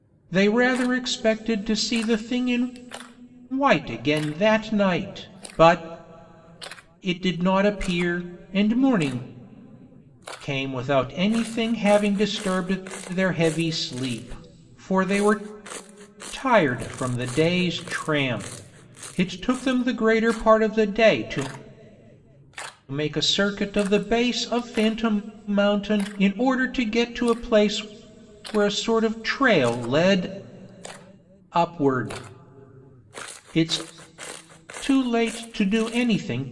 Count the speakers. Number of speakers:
1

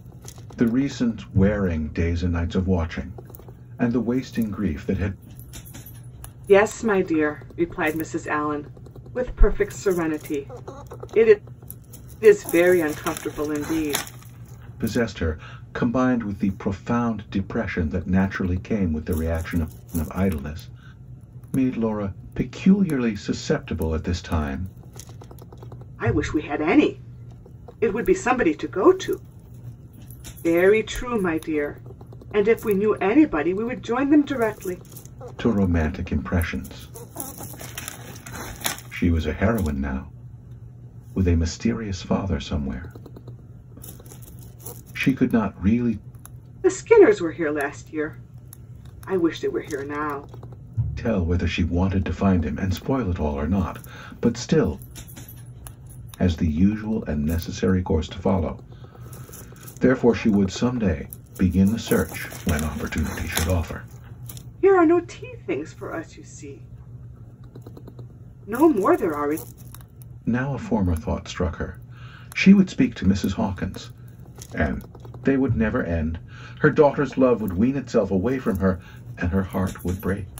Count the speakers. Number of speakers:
2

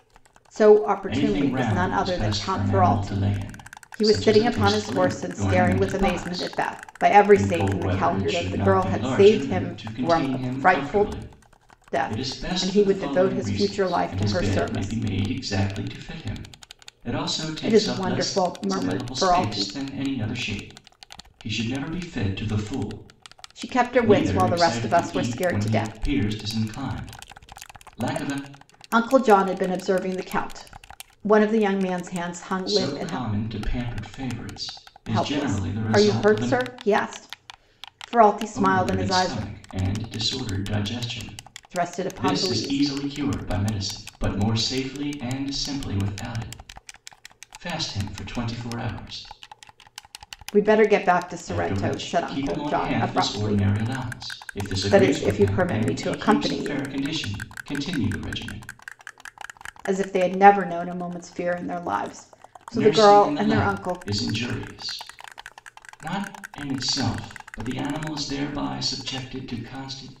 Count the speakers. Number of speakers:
2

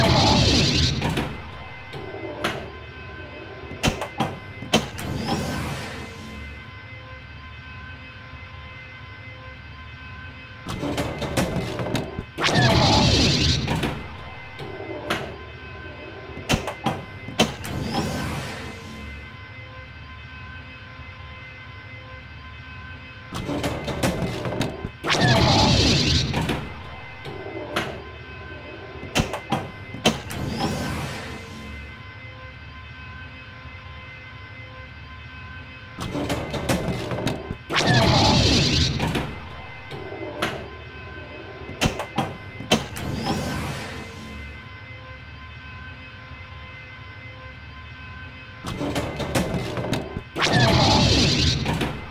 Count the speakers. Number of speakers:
0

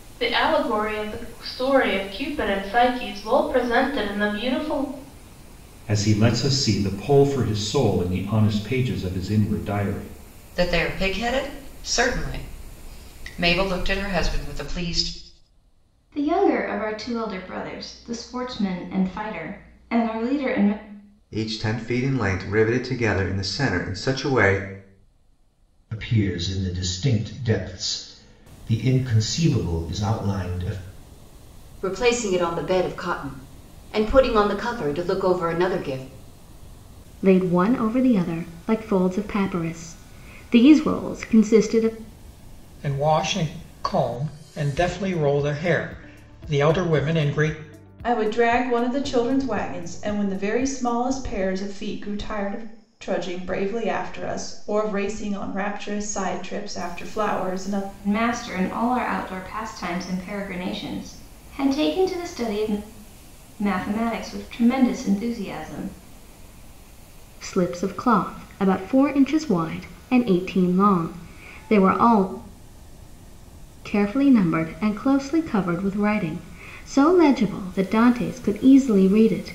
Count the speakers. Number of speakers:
10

